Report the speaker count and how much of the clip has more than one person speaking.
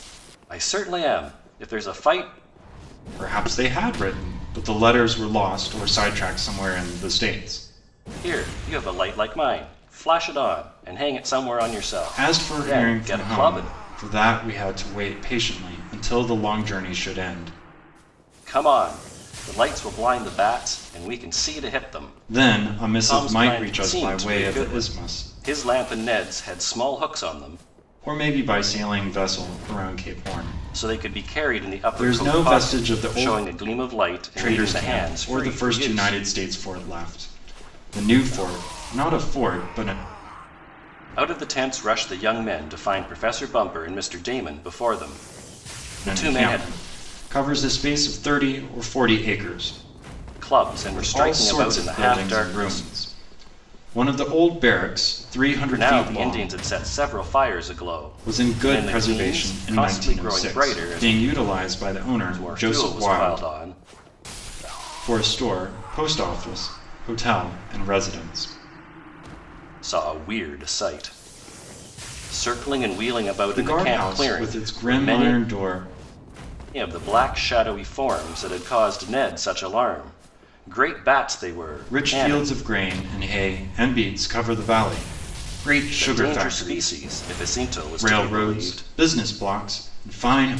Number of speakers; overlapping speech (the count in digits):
2, about 23%